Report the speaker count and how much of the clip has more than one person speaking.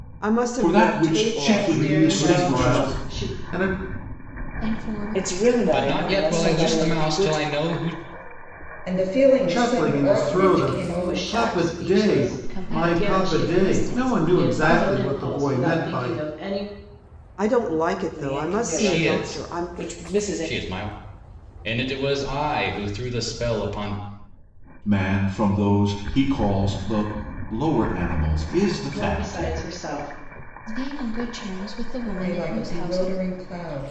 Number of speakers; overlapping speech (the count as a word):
eight, about 46%